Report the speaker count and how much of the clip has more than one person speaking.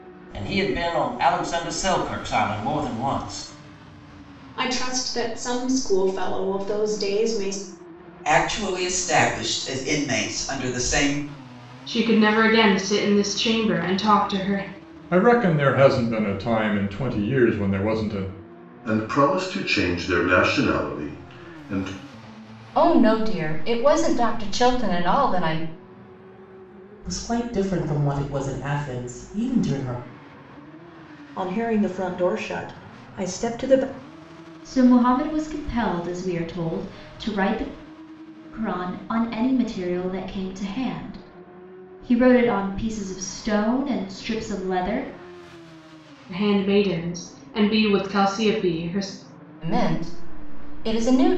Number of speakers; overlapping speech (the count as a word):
ten, no overlap